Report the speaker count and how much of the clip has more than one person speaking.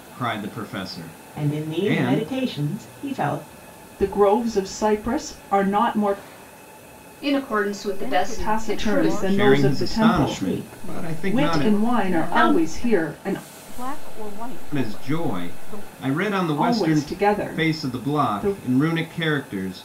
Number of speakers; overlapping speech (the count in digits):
5, about 45%